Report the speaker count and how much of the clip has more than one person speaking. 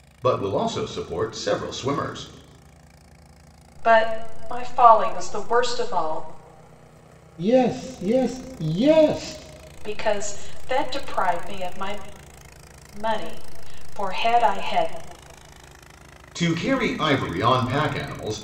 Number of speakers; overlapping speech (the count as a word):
three, no overlap